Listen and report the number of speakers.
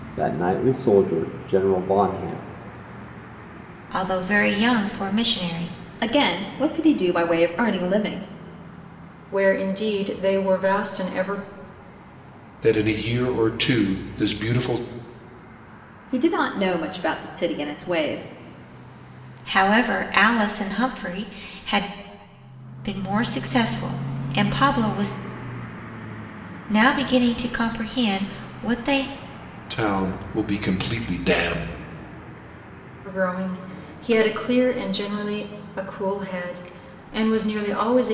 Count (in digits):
5